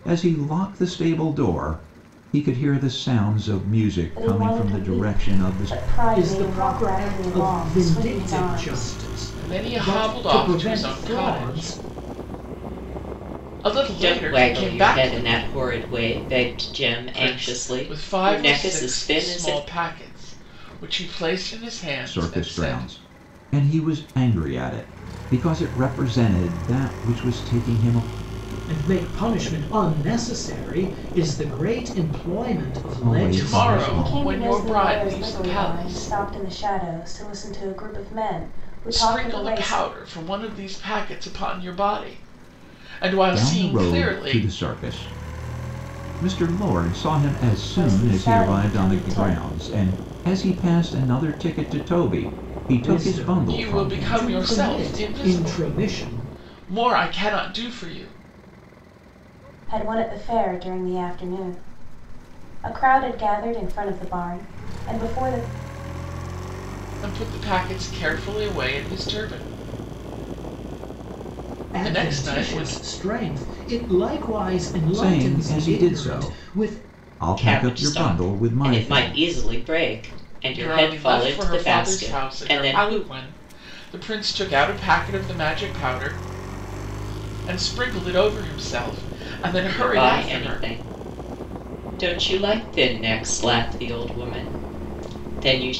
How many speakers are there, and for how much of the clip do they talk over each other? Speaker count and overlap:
five, about 32%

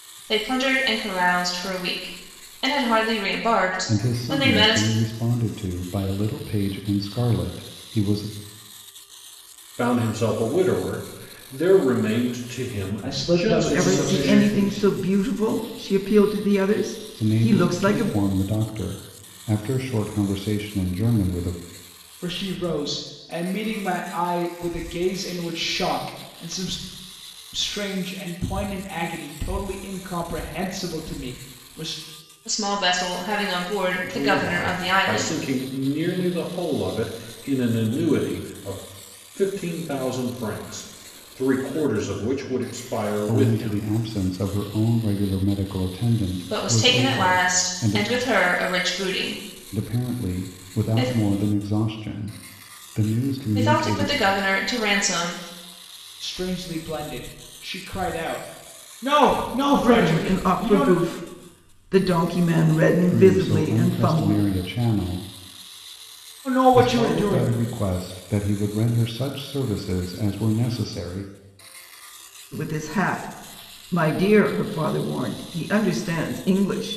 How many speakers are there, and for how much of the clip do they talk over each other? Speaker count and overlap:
five, about 17%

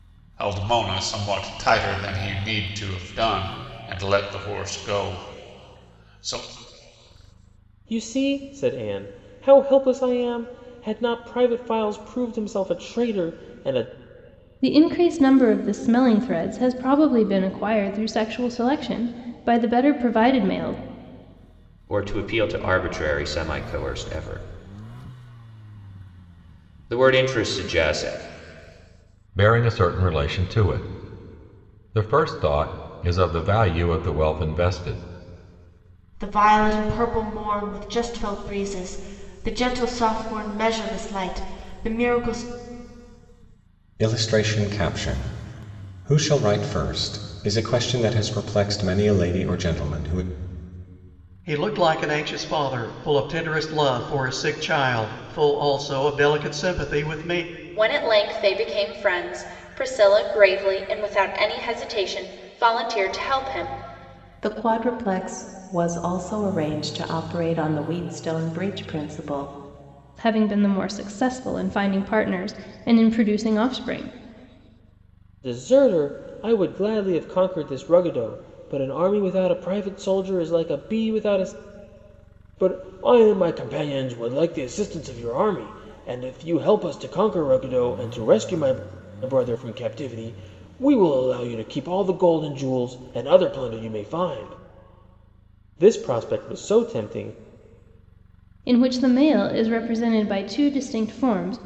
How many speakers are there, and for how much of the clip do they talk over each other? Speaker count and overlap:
ten, no overlap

